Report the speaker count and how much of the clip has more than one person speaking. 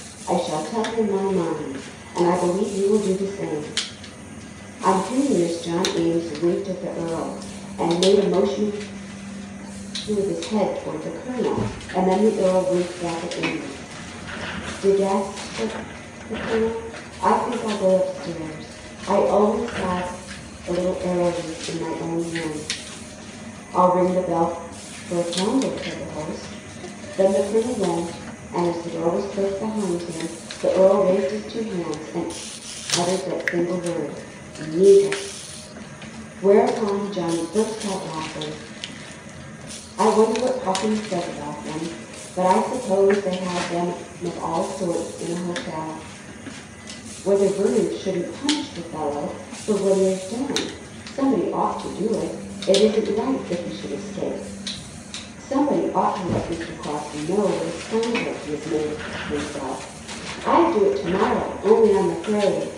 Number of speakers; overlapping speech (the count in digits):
1, no overlap